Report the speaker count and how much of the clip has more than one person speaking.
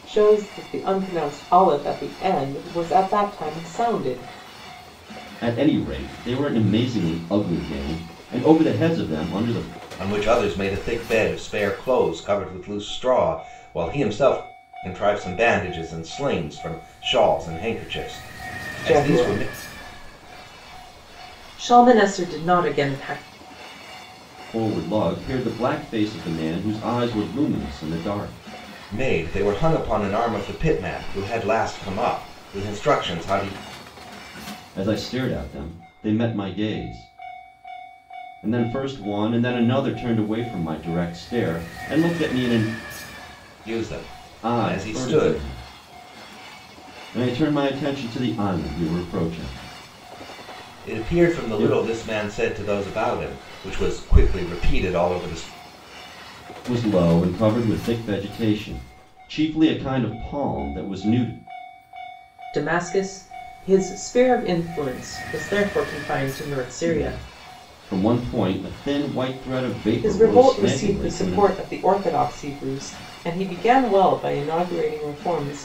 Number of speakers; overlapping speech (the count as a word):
three, about 6%